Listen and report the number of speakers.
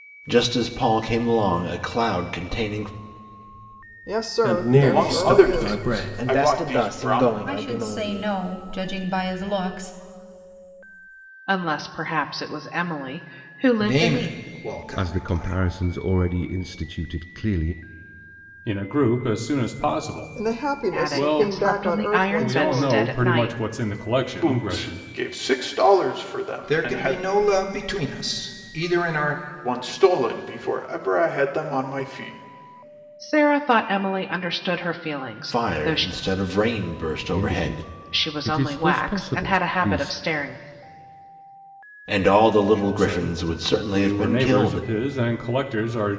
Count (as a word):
ten